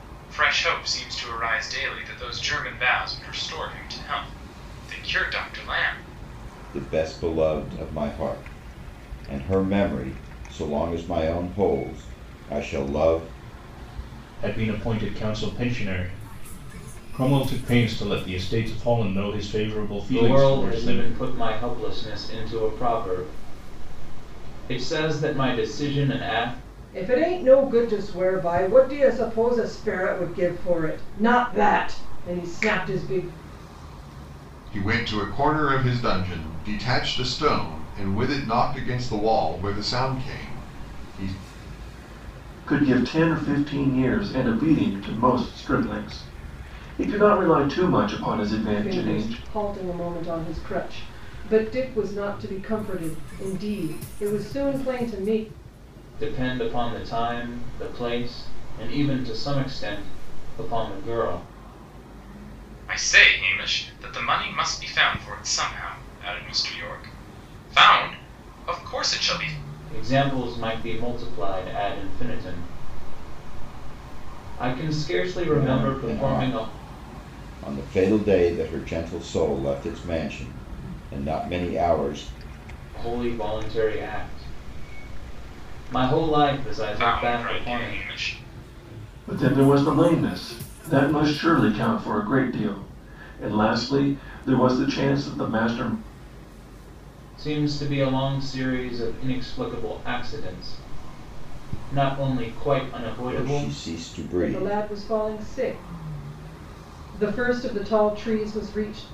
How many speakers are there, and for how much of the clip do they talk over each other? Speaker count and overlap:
seven, about 5%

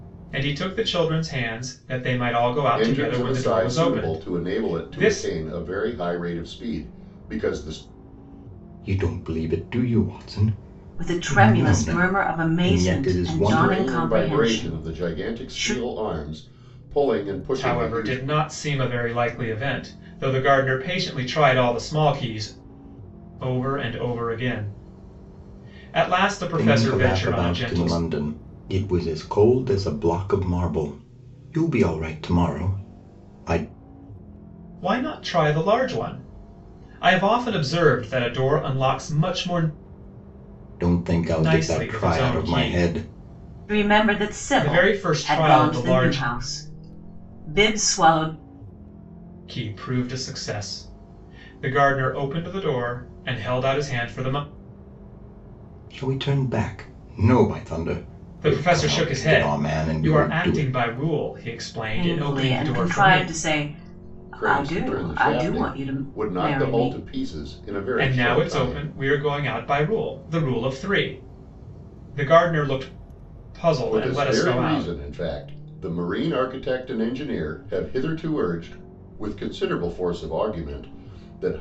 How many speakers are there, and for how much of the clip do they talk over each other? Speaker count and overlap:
four, about 28%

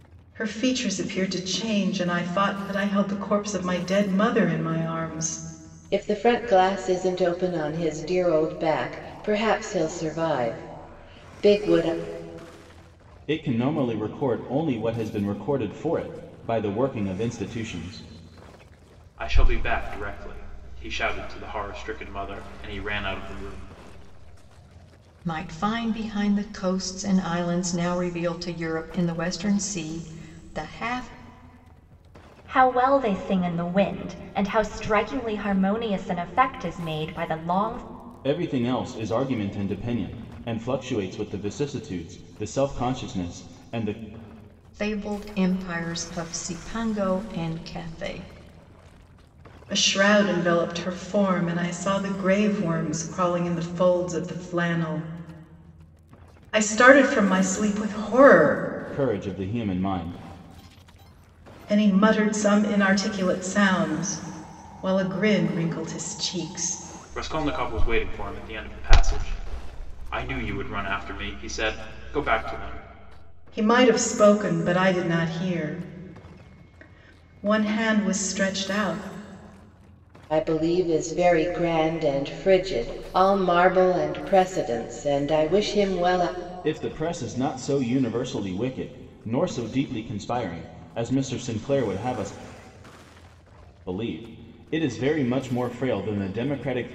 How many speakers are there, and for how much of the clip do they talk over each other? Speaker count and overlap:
six, no overlap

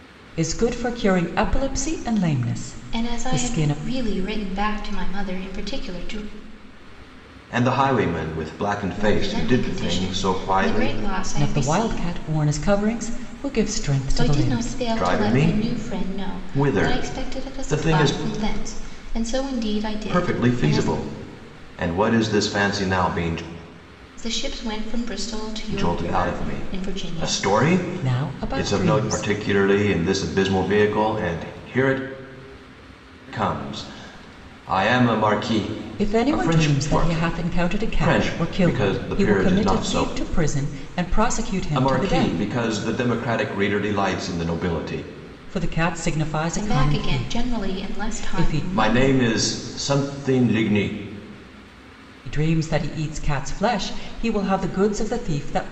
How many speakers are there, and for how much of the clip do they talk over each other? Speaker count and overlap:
three, about 34%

